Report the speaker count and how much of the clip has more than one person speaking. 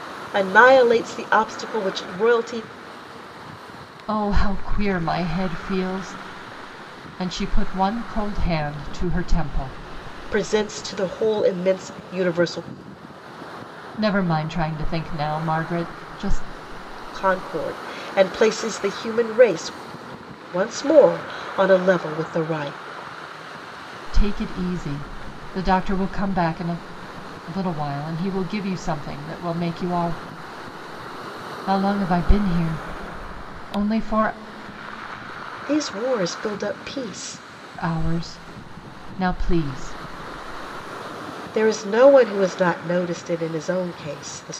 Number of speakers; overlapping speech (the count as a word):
two, no overlap